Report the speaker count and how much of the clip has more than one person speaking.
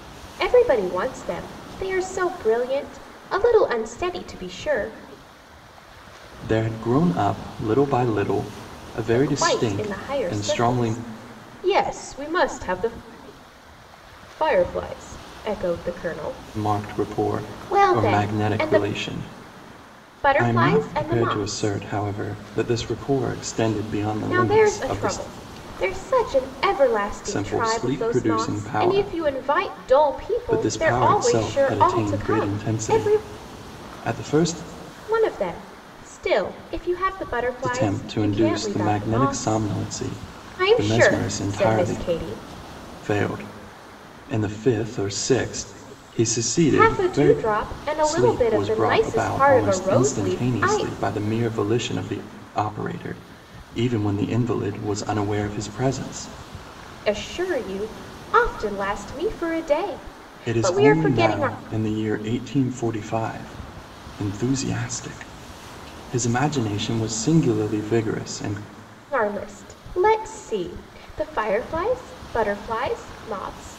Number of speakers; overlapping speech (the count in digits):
2, about 27%